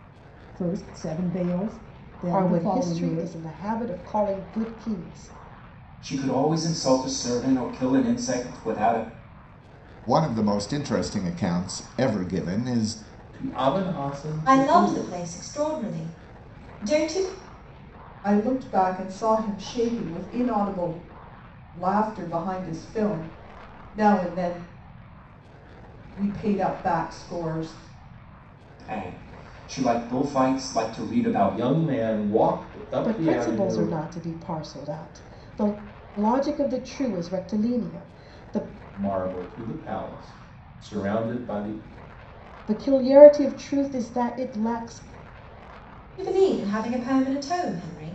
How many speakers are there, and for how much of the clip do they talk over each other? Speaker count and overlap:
seven, about 6%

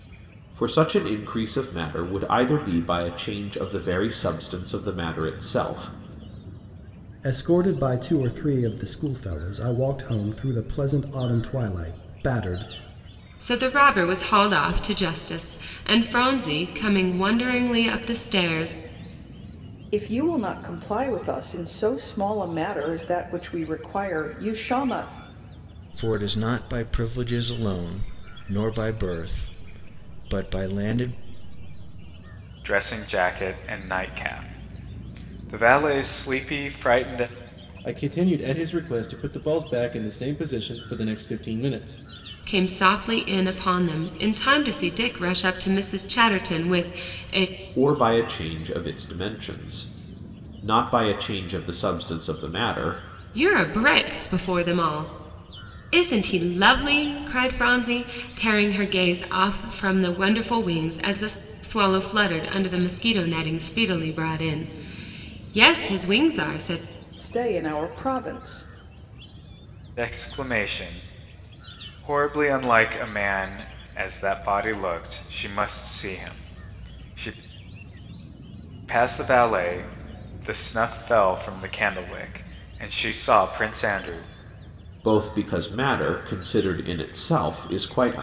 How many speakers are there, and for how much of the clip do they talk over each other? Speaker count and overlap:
seven, no overlap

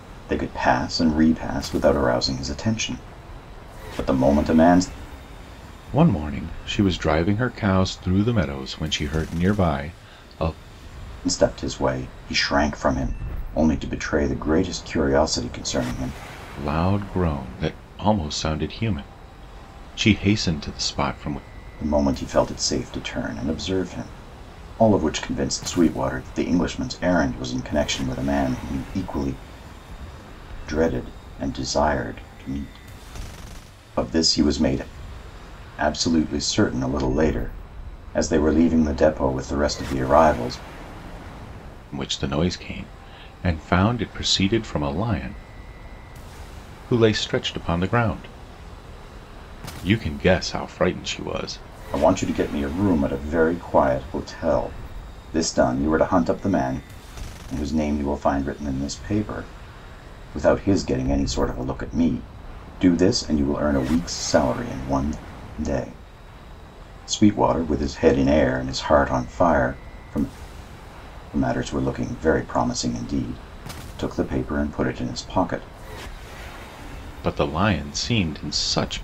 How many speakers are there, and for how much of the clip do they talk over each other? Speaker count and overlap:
two, no overlap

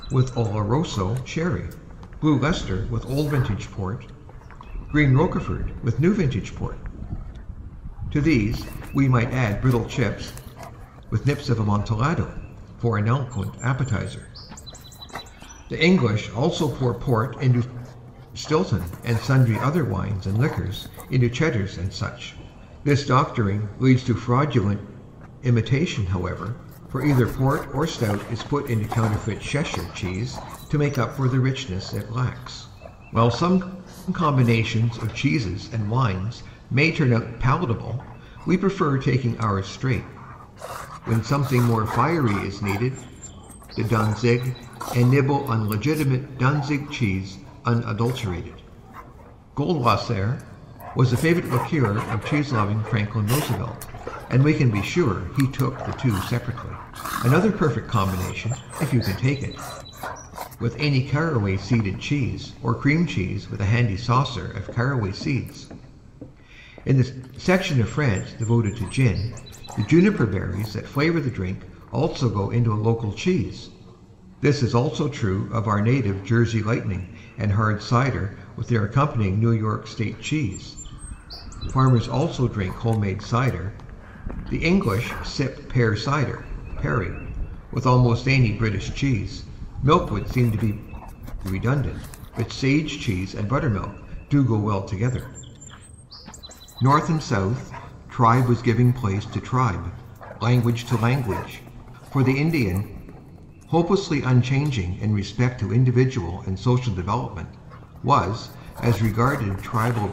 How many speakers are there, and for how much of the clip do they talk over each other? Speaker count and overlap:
one, no overlap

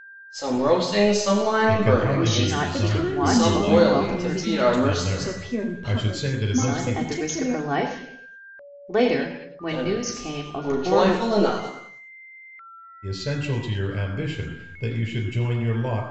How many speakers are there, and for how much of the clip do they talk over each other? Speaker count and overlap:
four, about 47%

